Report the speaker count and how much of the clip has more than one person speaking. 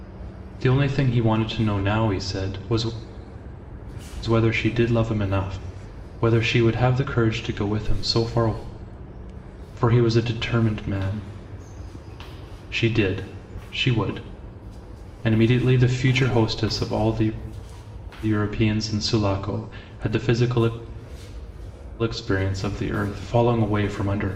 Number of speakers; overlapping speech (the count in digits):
1, no overlap